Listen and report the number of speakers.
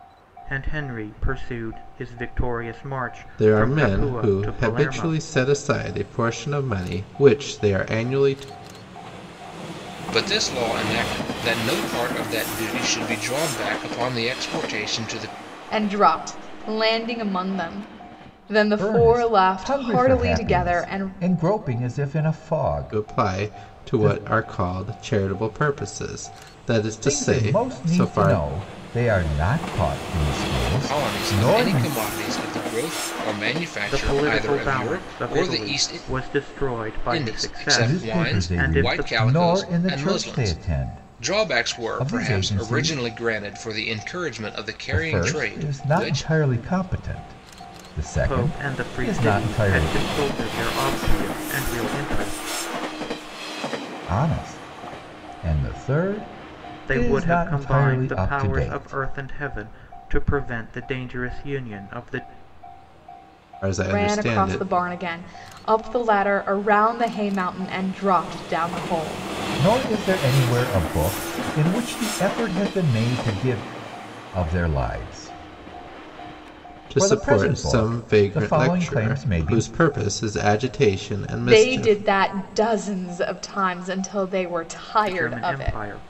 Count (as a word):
five